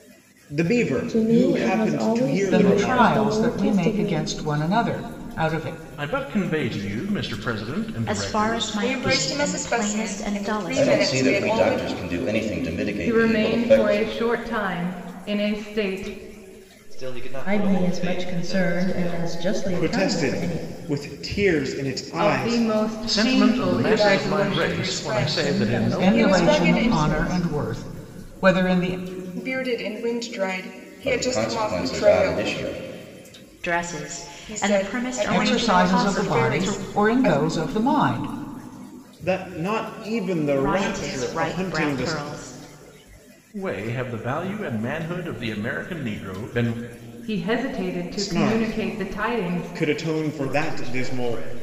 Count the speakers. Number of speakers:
ten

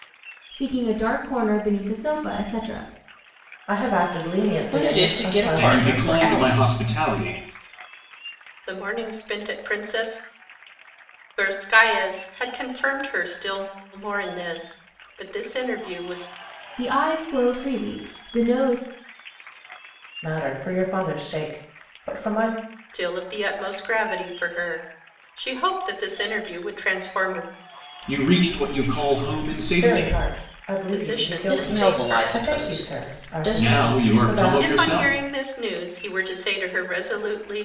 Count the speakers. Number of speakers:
five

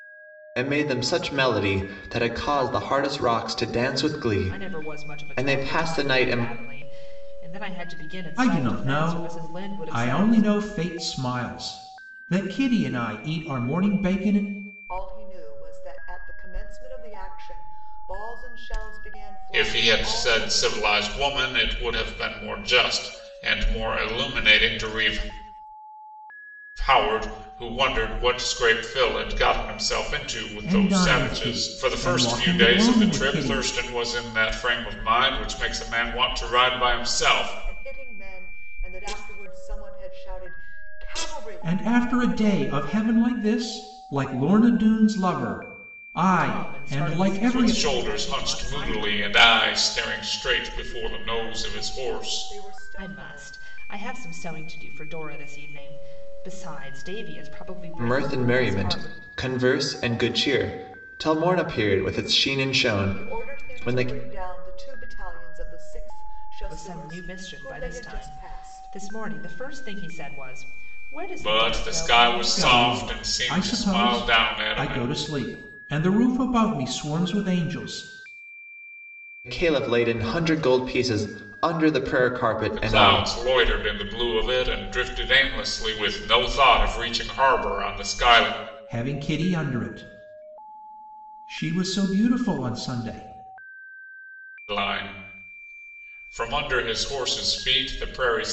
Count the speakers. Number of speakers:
five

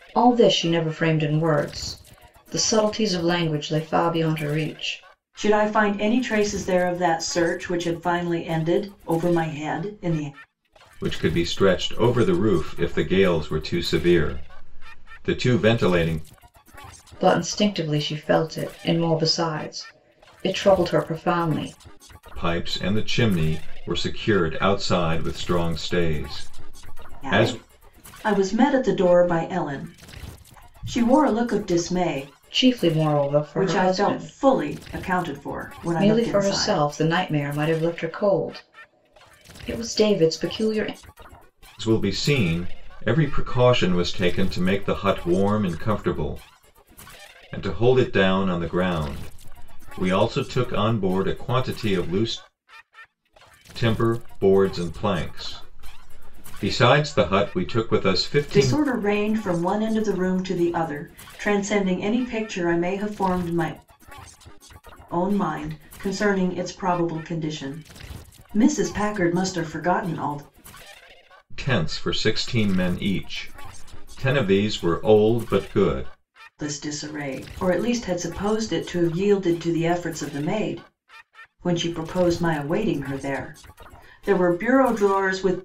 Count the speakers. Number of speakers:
three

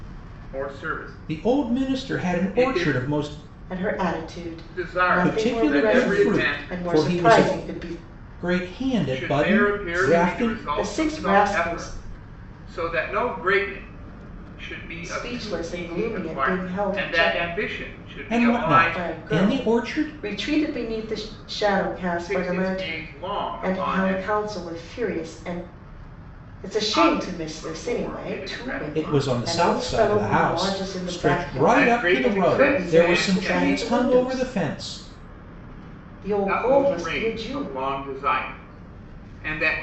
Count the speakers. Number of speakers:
three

